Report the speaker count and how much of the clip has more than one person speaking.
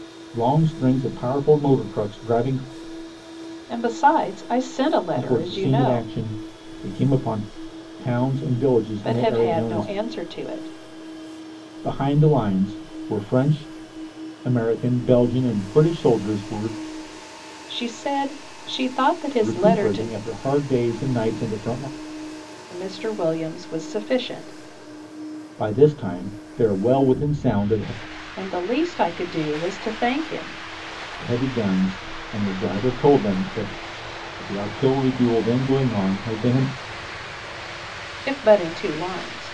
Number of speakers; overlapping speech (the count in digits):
2, about 7%